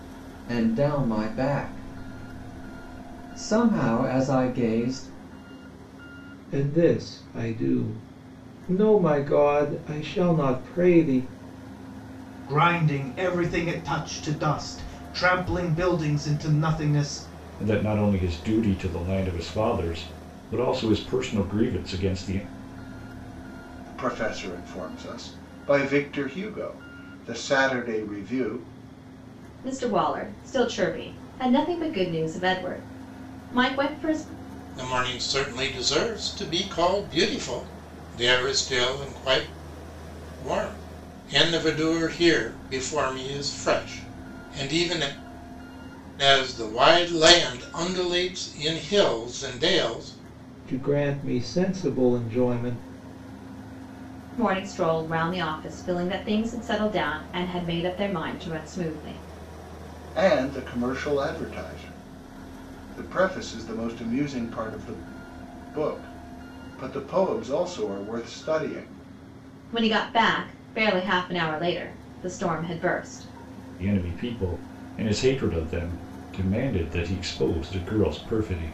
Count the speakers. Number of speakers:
7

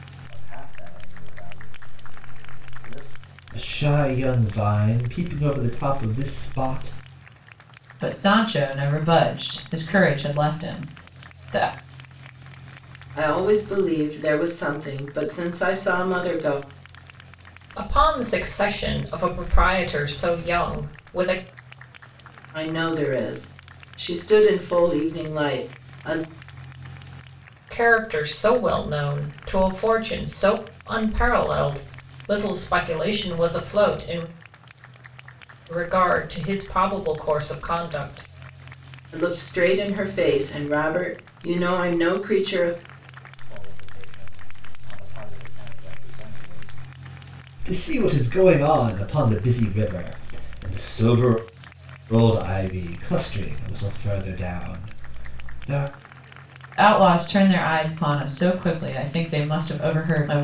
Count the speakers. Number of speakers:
5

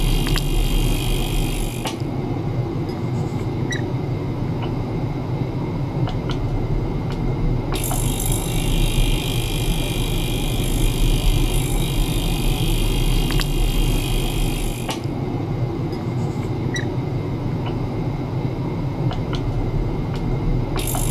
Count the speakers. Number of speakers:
0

